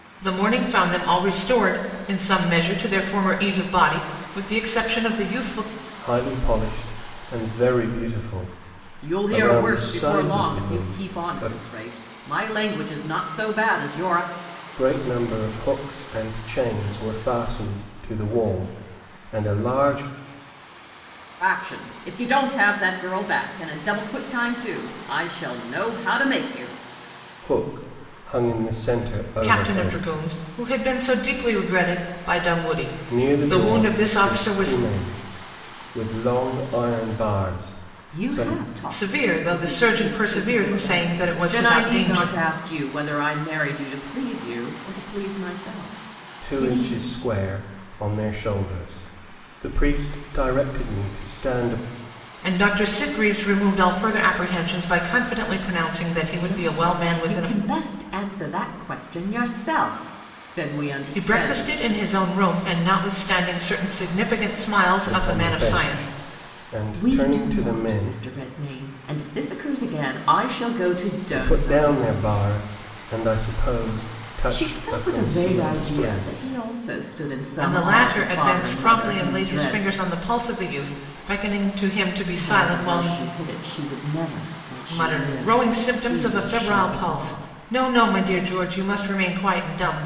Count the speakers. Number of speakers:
three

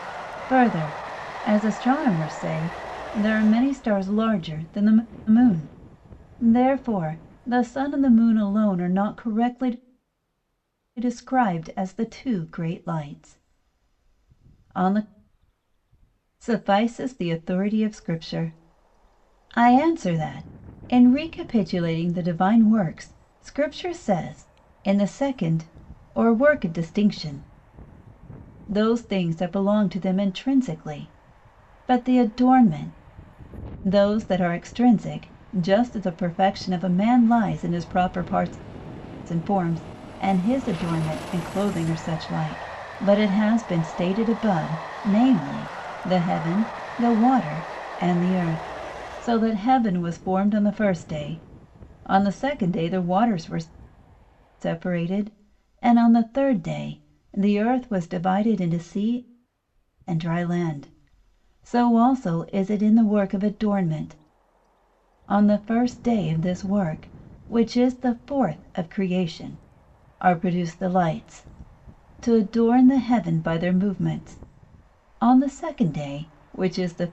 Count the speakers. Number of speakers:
one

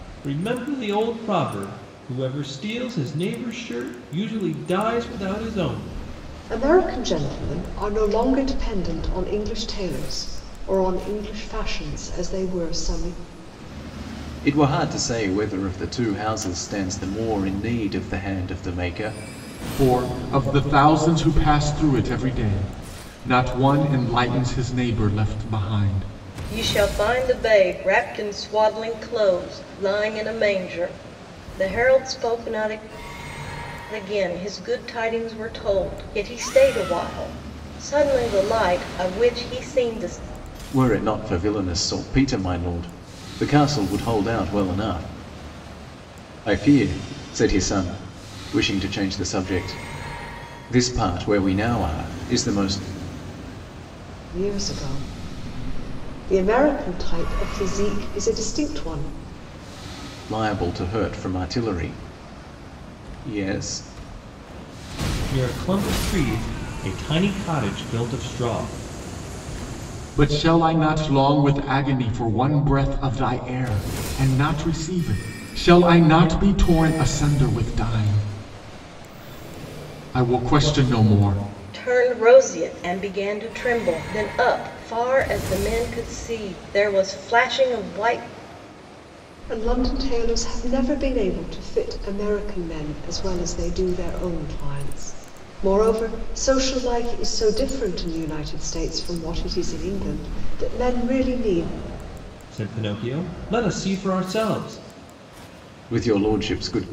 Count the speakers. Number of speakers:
five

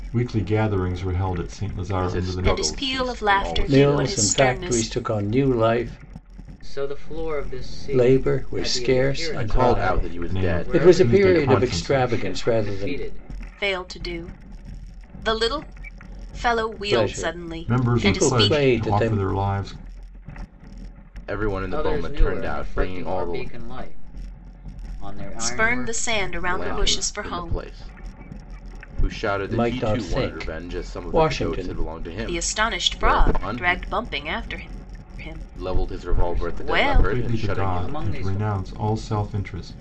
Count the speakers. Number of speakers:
five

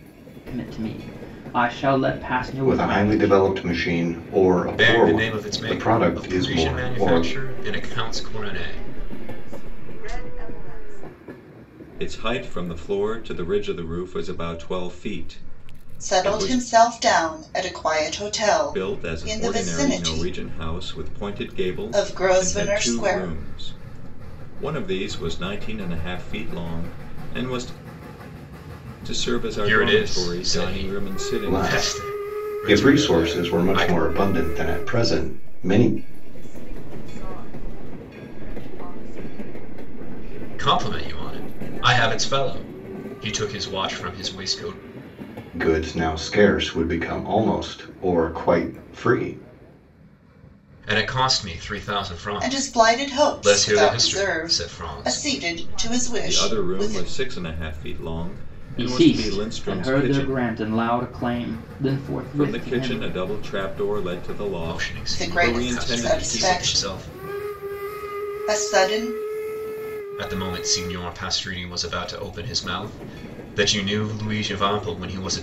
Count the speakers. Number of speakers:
six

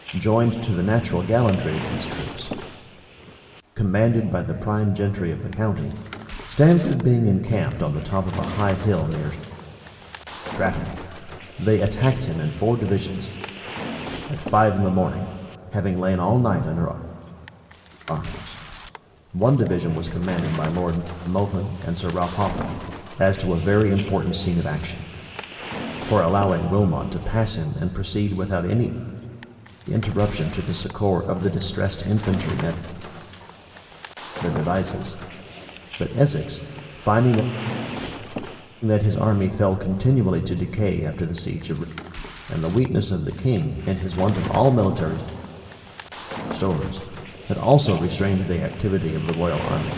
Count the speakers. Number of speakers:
one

